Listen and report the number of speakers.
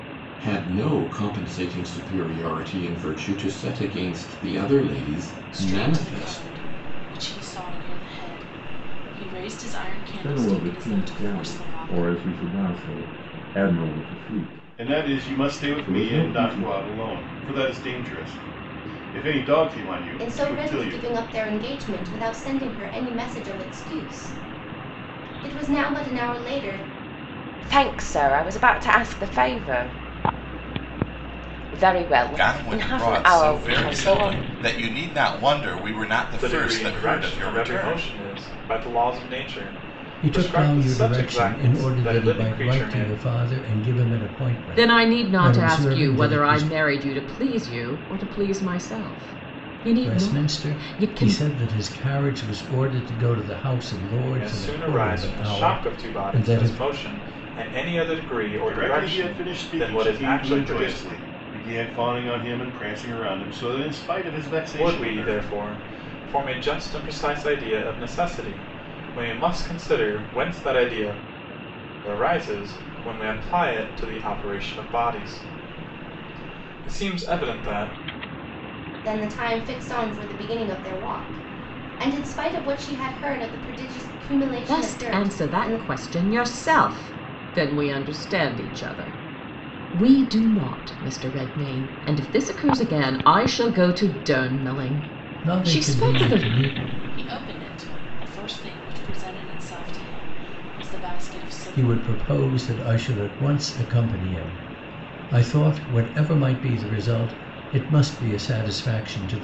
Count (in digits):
10